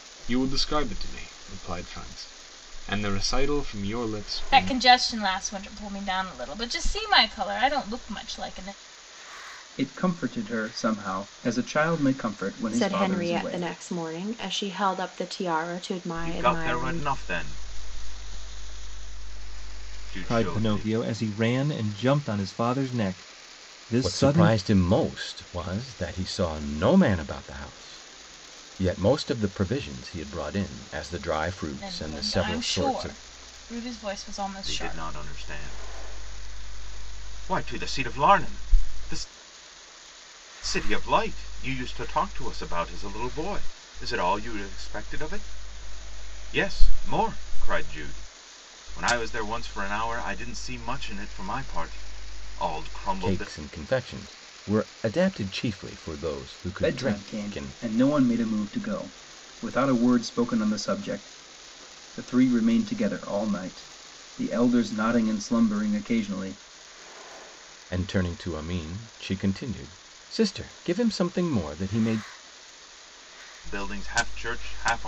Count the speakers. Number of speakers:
7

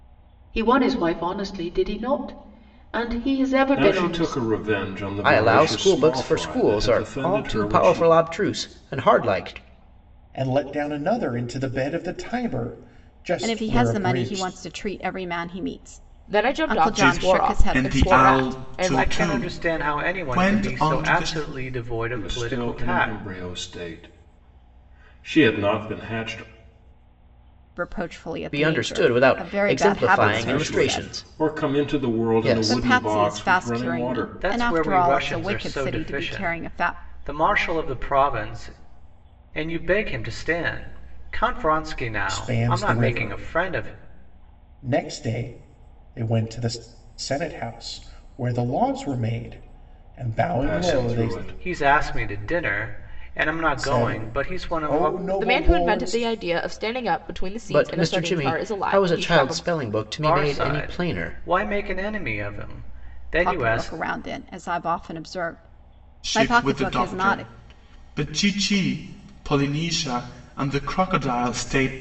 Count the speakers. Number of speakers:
8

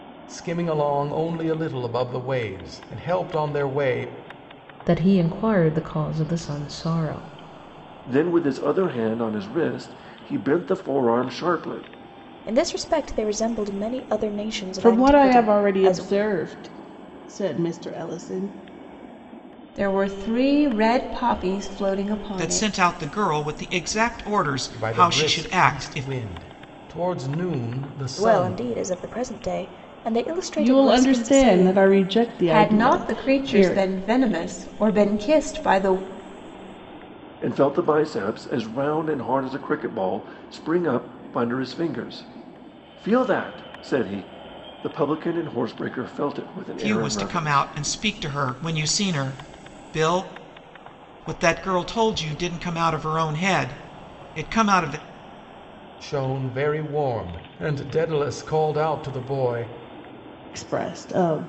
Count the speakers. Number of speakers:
7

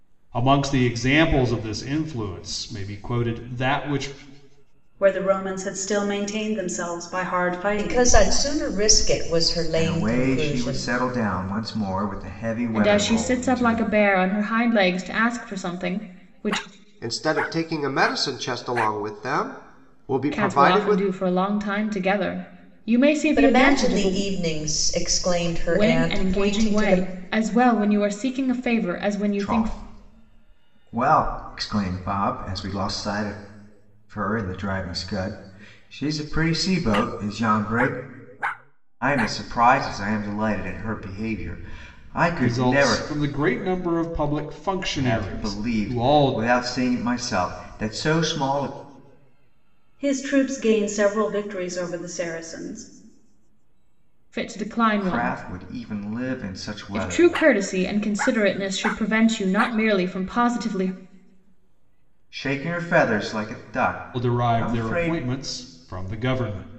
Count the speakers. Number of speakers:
6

